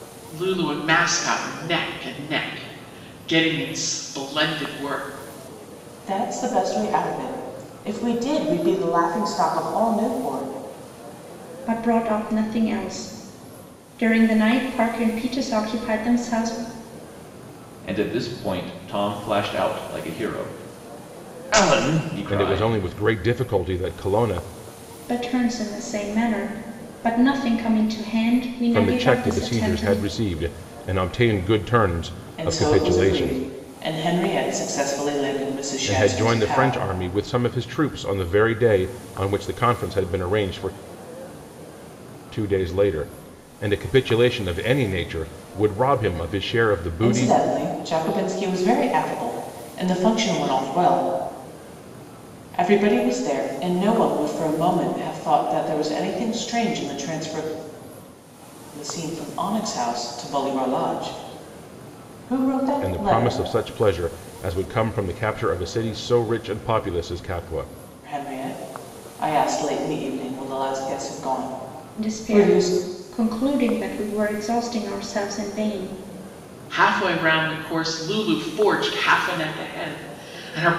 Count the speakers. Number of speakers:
5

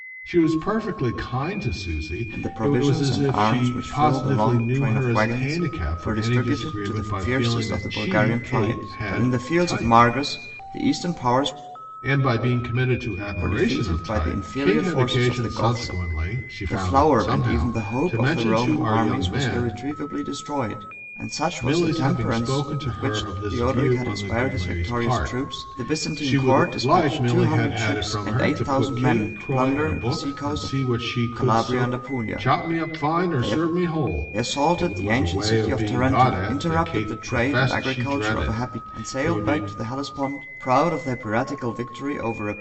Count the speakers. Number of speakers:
2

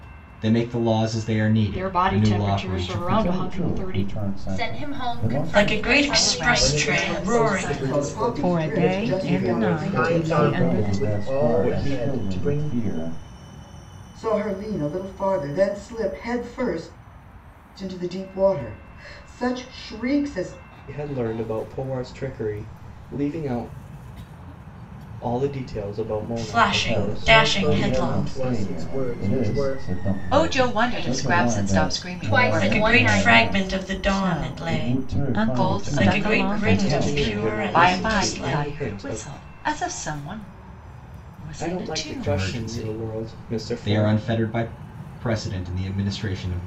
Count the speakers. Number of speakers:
10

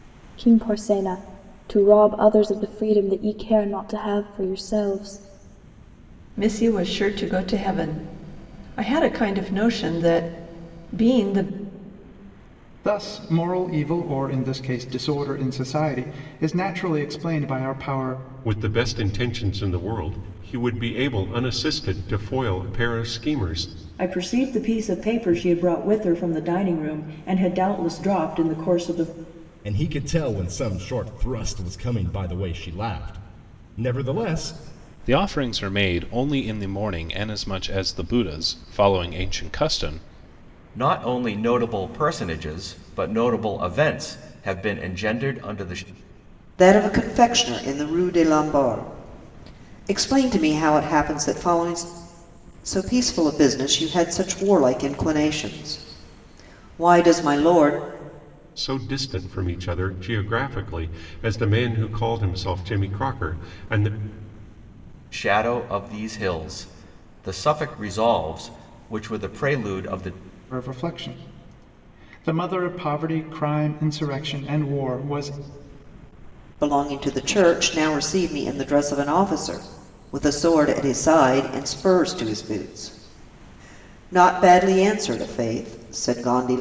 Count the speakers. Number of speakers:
9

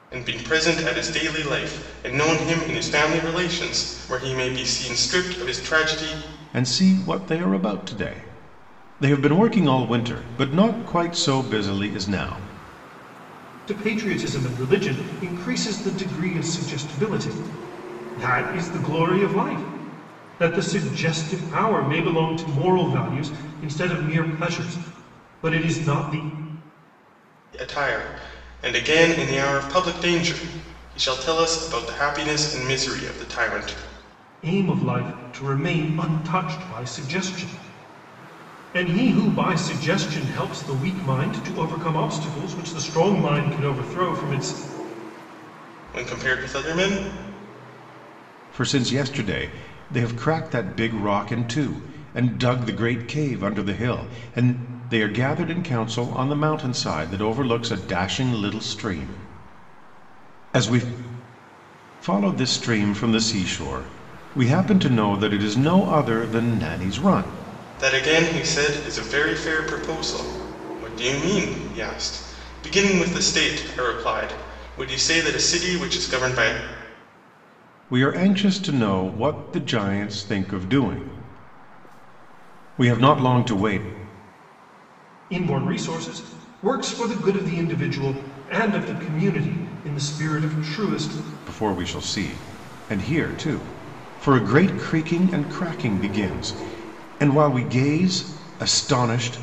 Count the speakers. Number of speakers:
3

